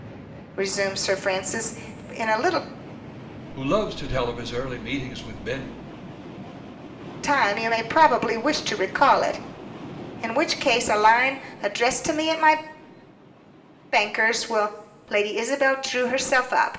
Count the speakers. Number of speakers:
2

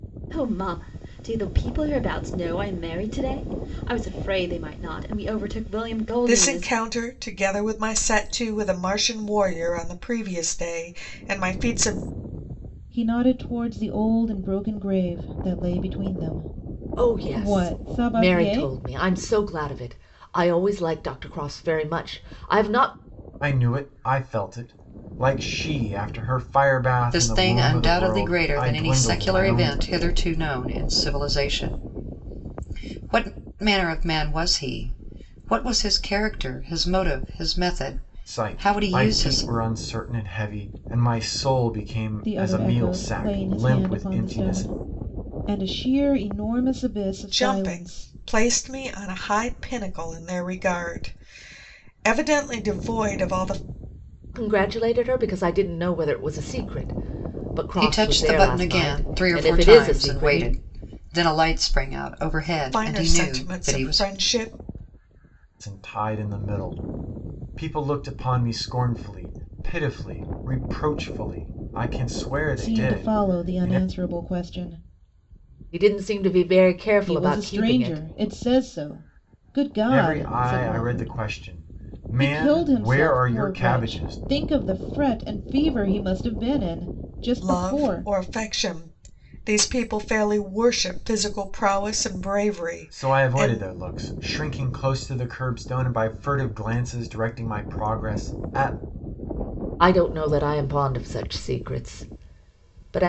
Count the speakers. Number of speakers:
6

